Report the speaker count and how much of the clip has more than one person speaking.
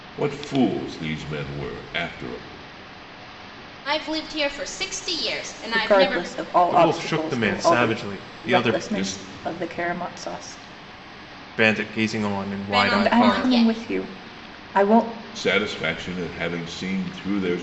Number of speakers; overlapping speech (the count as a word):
four, about 24%